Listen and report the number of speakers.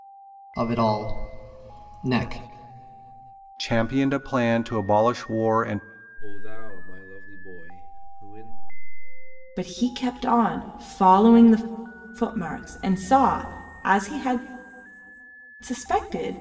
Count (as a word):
four